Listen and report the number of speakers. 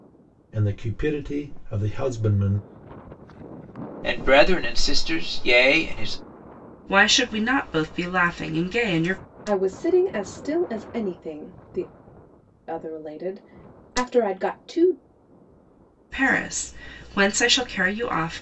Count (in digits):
4